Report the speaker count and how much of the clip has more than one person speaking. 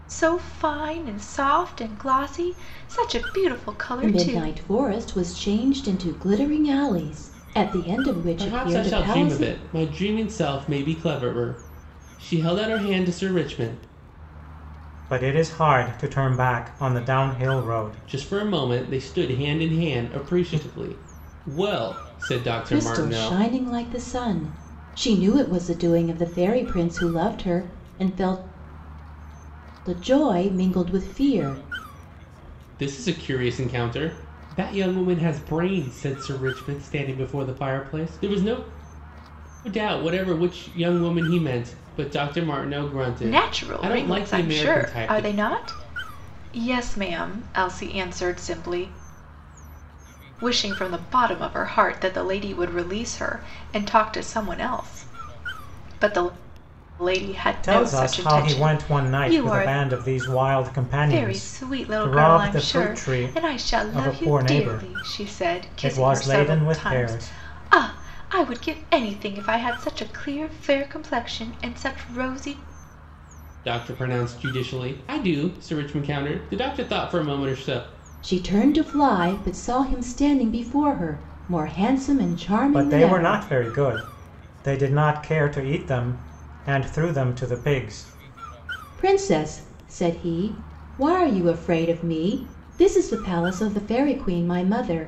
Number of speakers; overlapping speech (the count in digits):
4, about 17%